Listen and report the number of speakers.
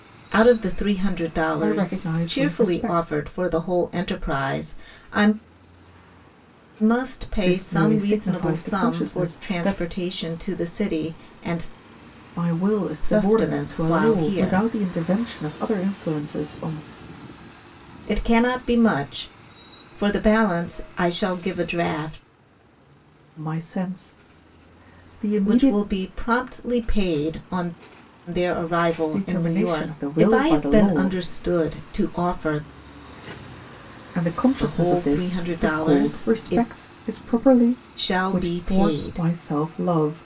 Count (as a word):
two